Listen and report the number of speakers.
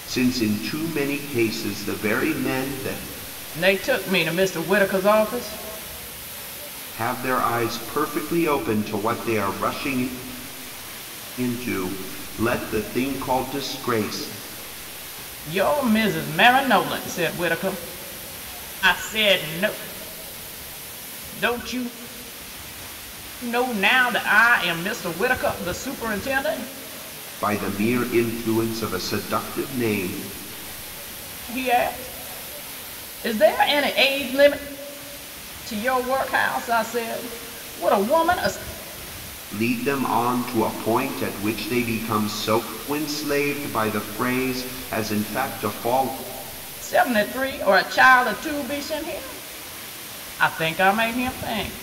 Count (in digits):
2